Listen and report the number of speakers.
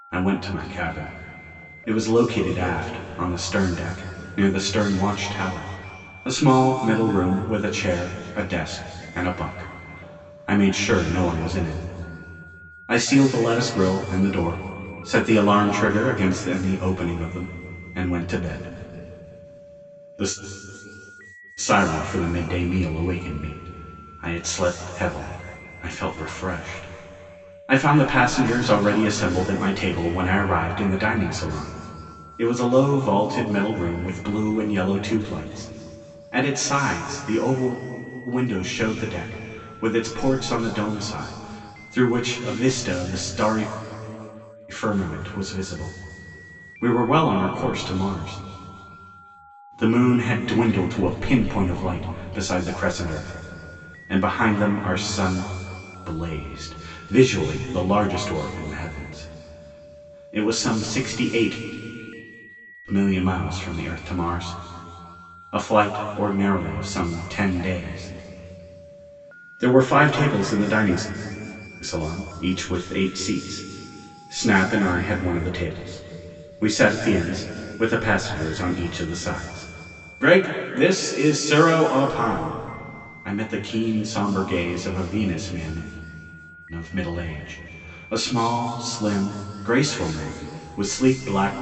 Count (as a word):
one